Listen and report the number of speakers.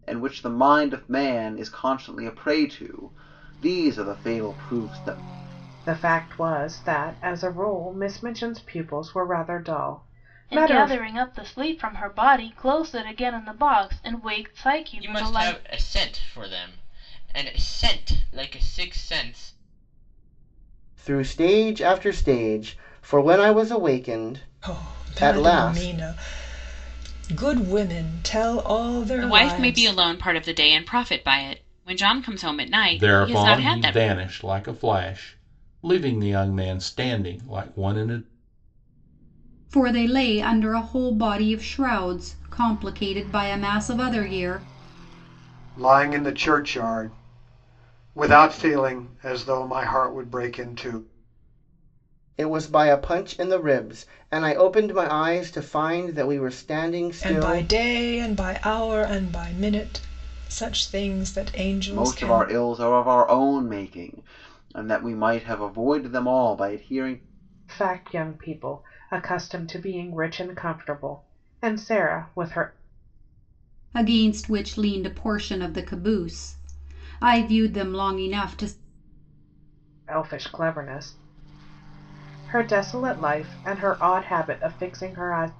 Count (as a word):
ten